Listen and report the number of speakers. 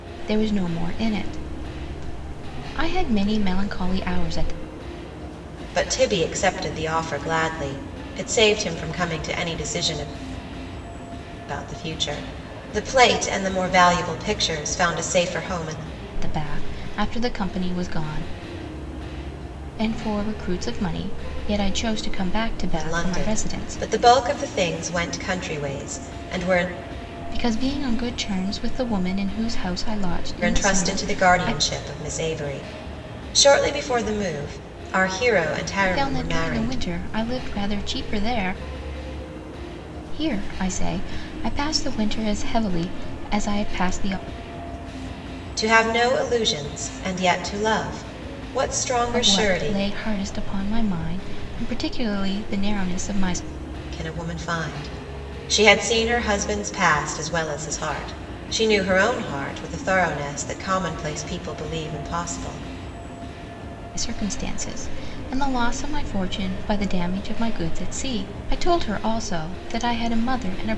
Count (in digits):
2